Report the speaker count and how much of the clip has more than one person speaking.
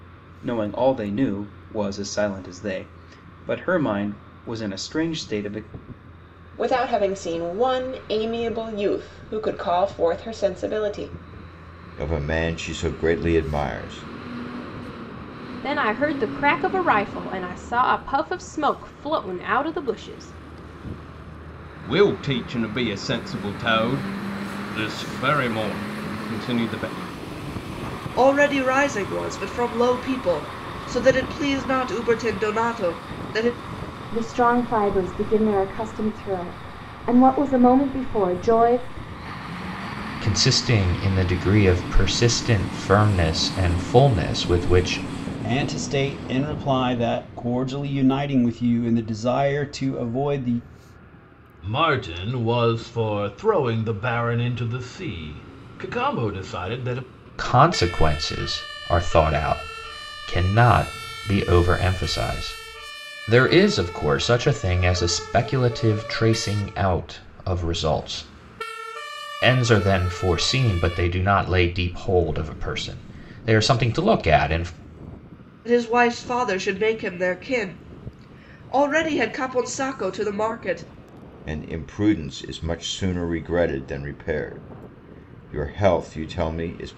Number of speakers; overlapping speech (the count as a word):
ten, no overlap